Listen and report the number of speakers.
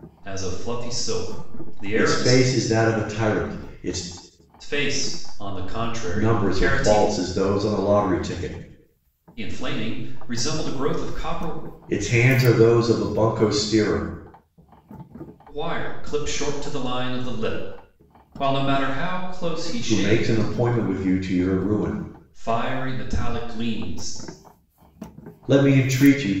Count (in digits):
2